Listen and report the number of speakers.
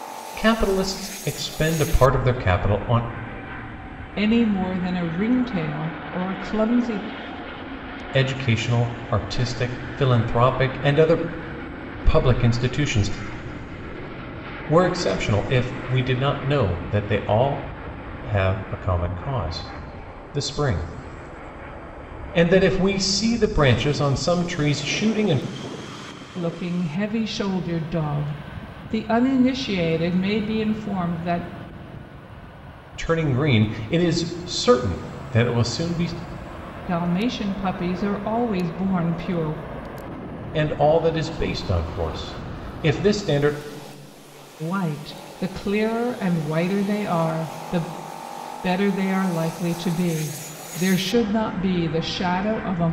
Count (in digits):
2